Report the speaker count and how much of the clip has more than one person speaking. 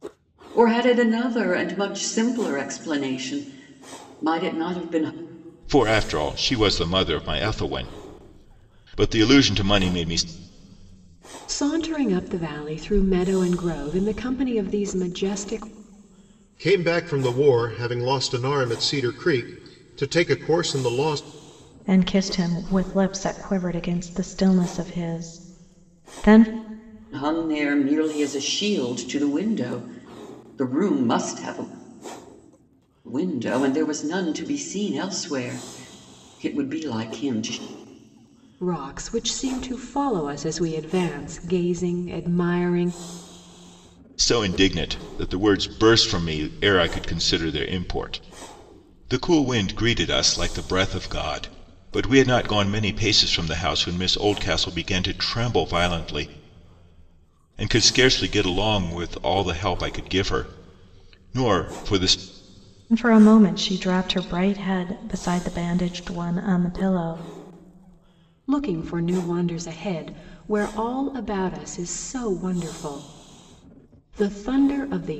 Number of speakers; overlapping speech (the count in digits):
5, no overlap